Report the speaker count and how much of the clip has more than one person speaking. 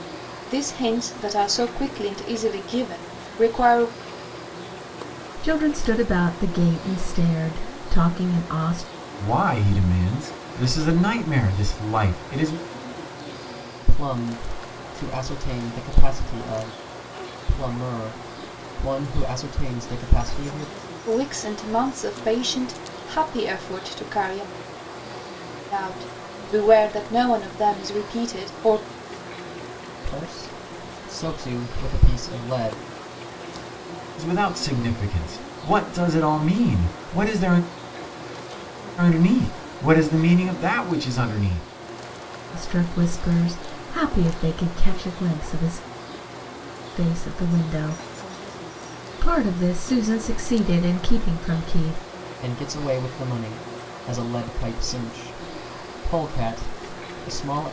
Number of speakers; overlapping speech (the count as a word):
four, no overlap